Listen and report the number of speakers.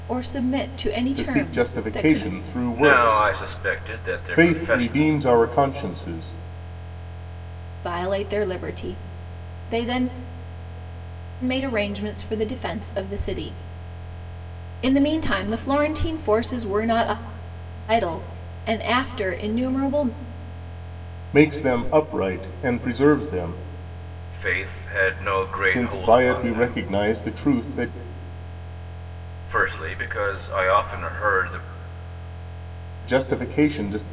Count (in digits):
3